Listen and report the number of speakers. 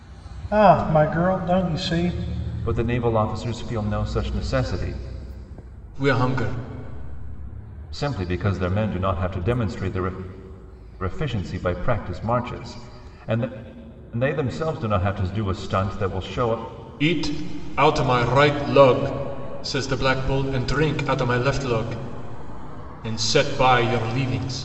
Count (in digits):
3